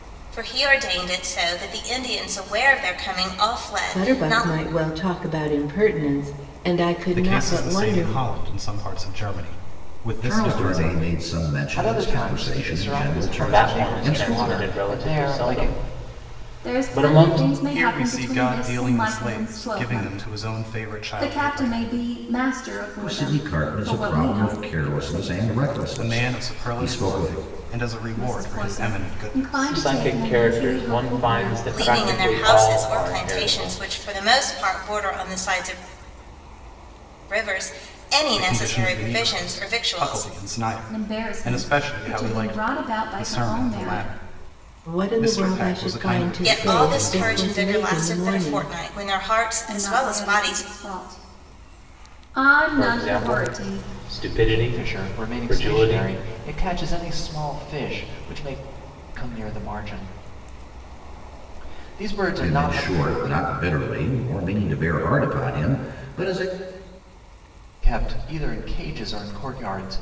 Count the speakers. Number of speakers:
seven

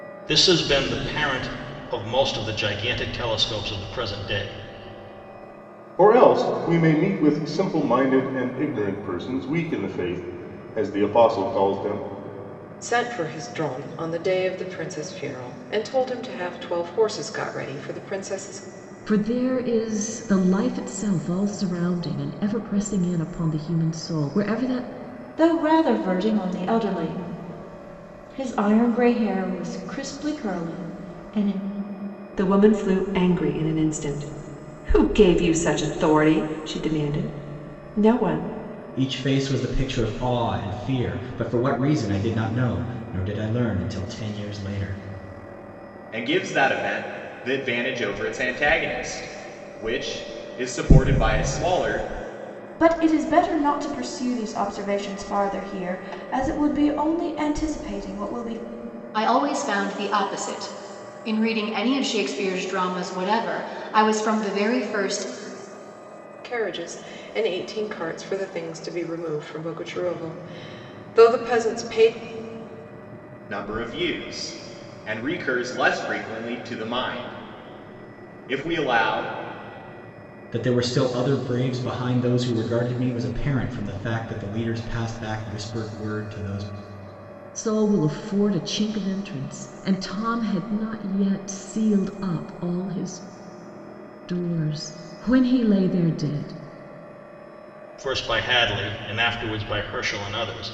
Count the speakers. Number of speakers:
ten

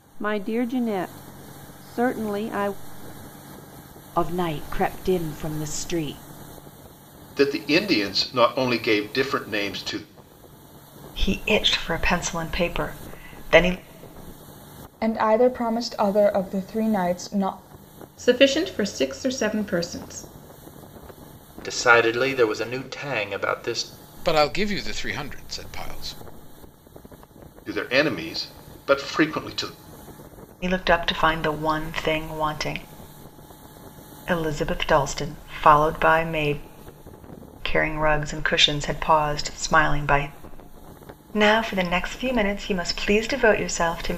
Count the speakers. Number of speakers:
eight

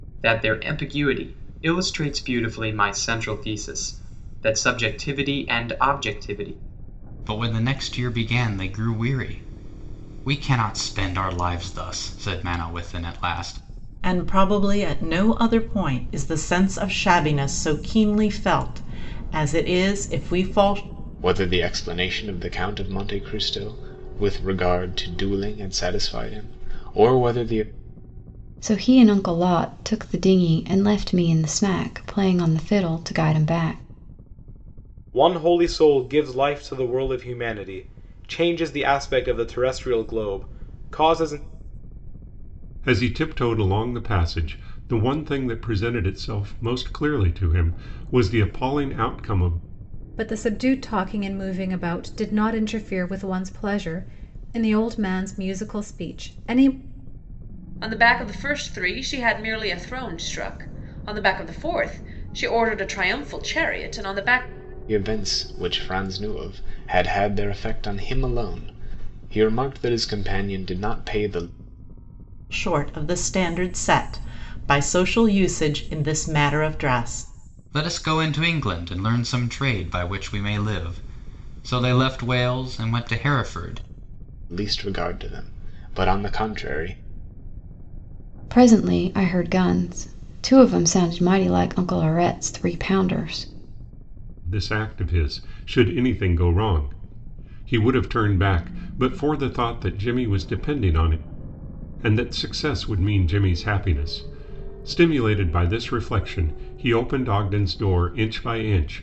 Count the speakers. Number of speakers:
nine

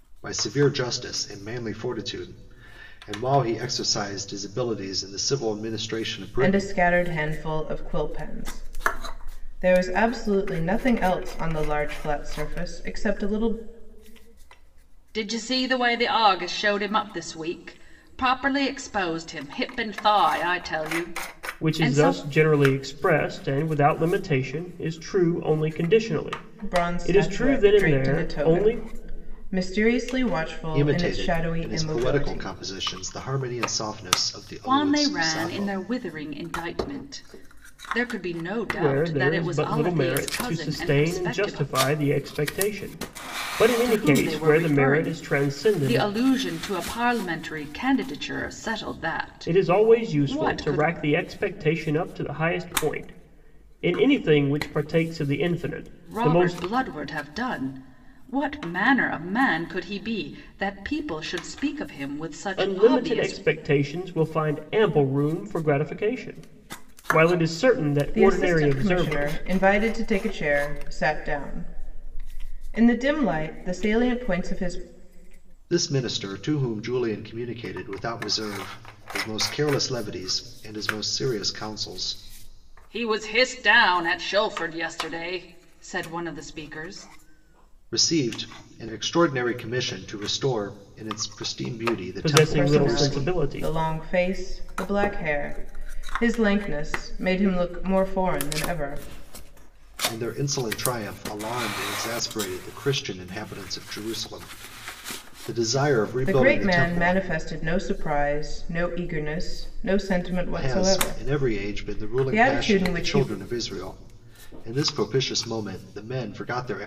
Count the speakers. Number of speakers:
four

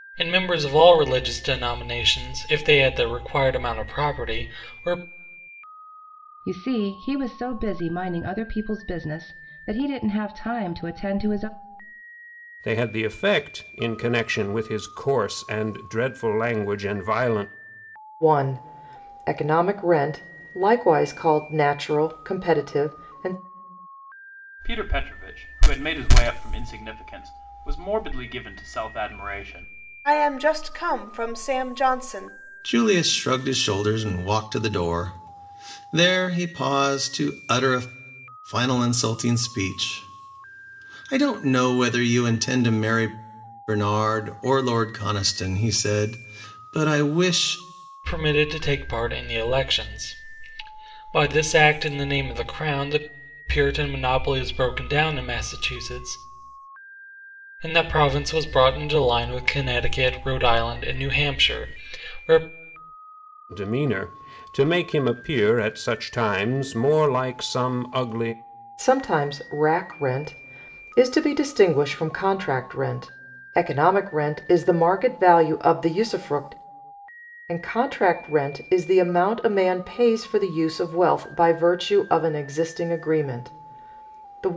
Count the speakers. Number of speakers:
seven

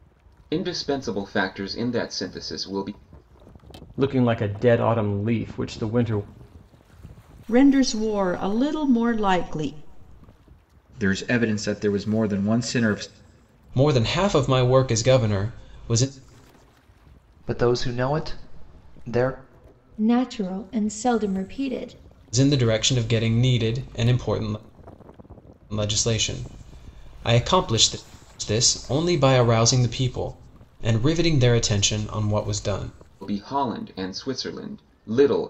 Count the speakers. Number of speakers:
seven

